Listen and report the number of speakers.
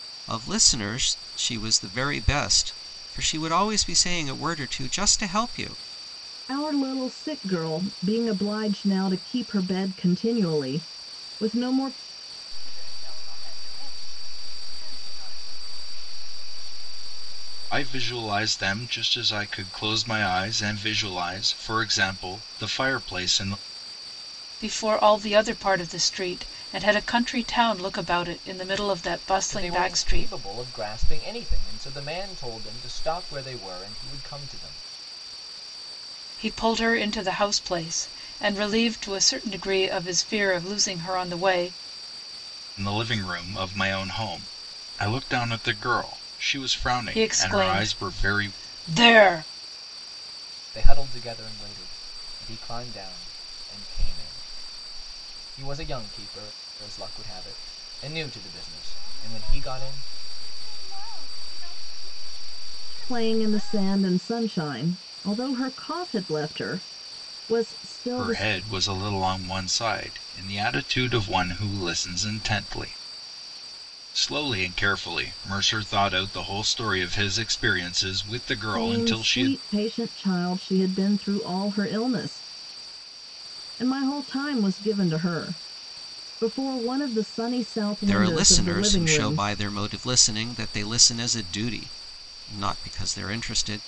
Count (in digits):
6